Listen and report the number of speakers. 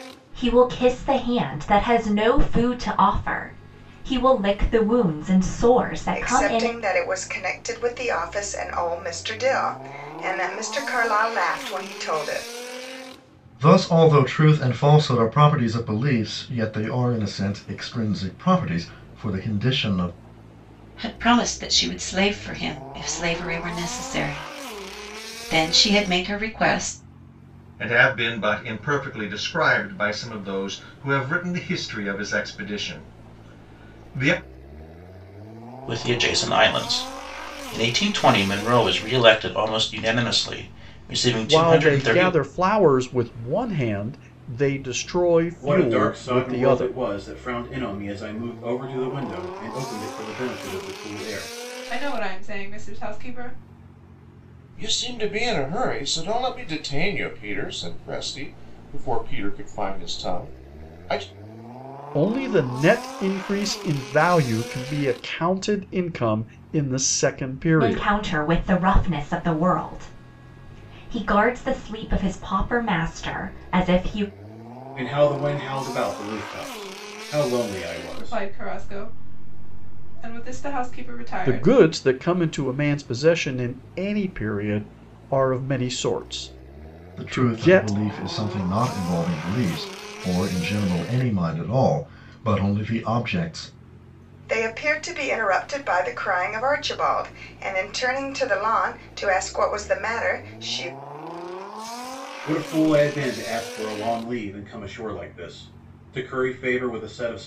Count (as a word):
ten